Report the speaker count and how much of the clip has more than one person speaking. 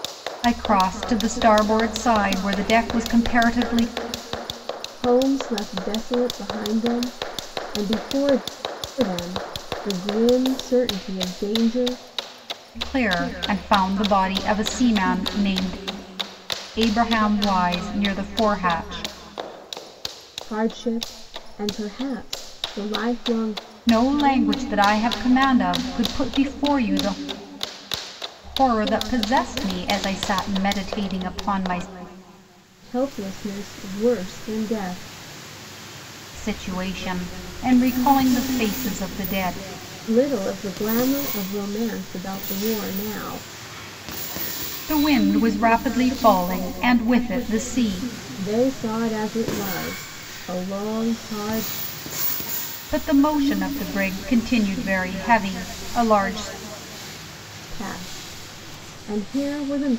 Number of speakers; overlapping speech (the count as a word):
two, no overlap